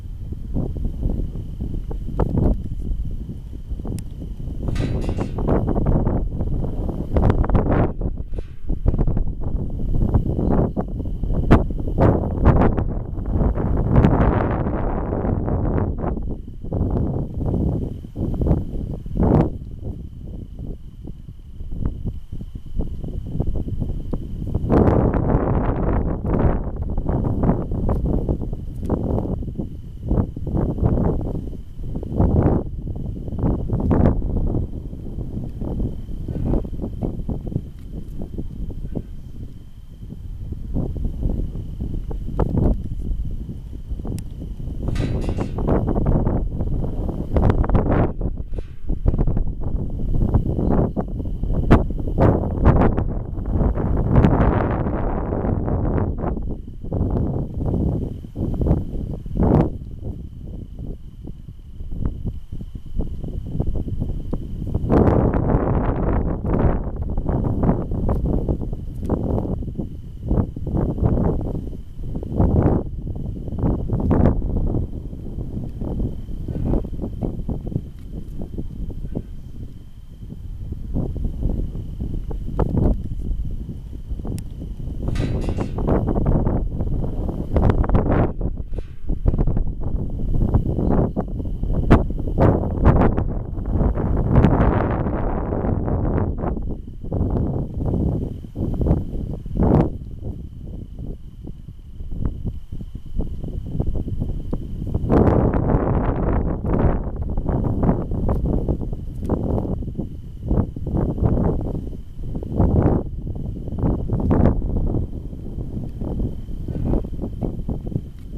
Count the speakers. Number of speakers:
zero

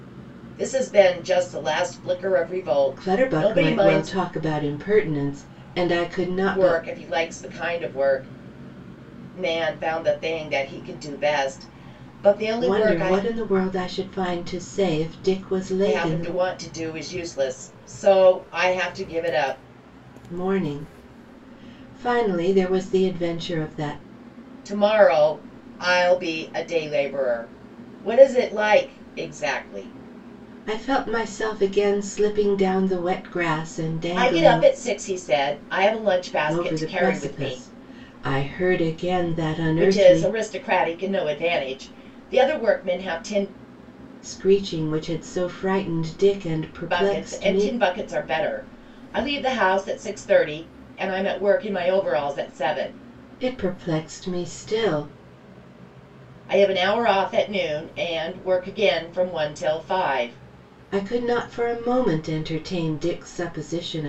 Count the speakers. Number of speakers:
two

